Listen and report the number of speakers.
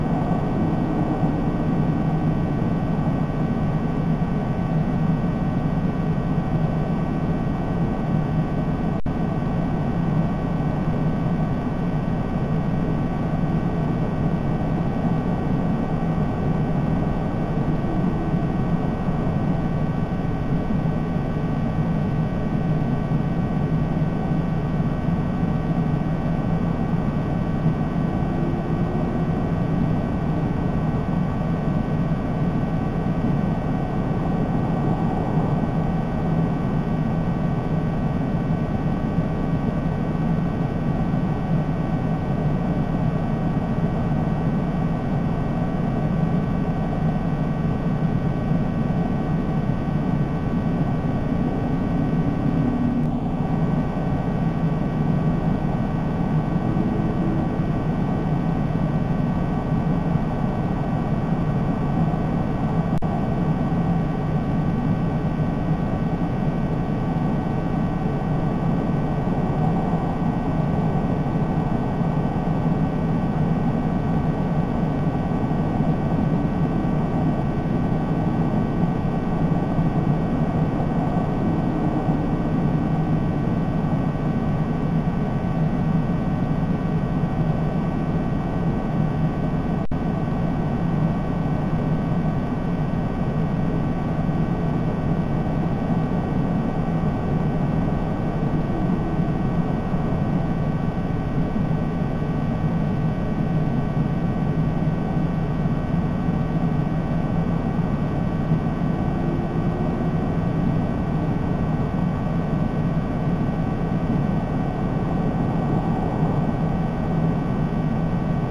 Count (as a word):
zero